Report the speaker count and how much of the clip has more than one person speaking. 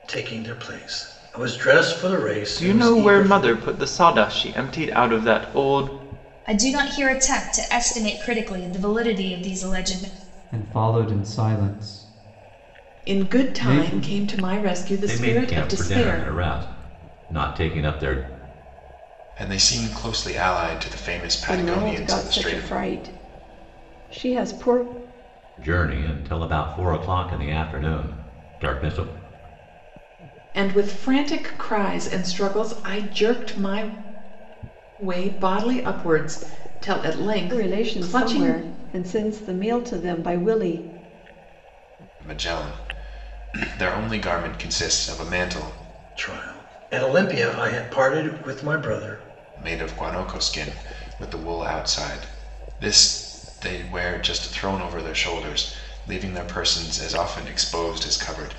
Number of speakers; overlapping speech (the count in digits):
8, about 10%